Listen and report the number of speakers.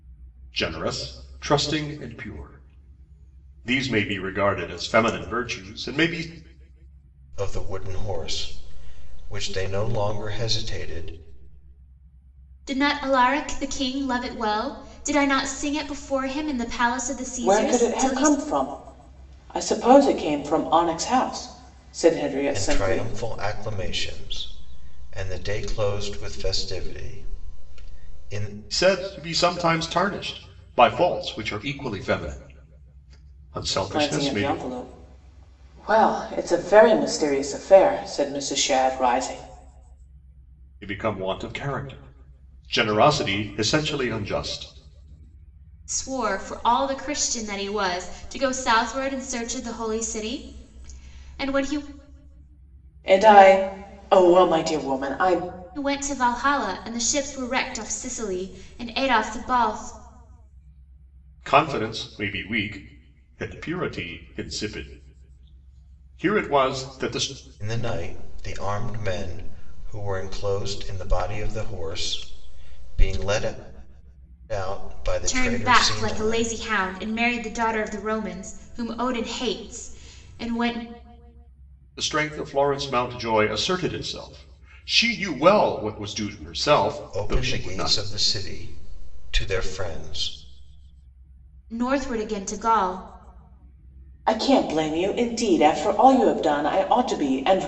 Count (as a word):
four